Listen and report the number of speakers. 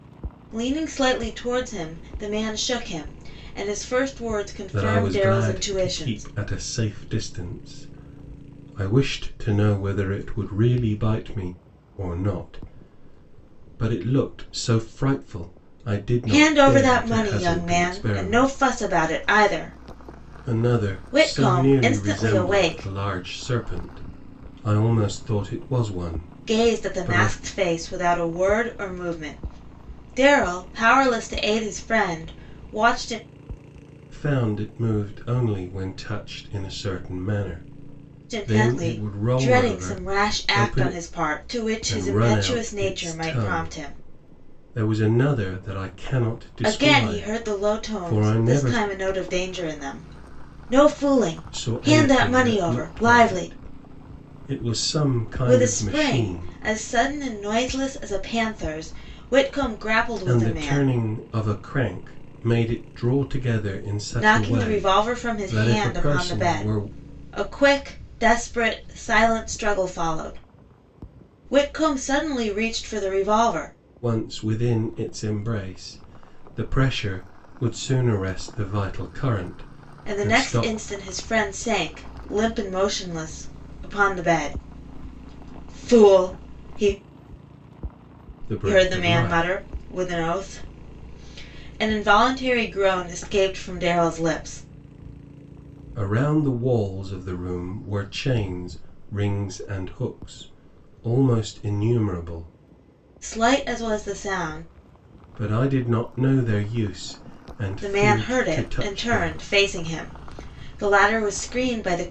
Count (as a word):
two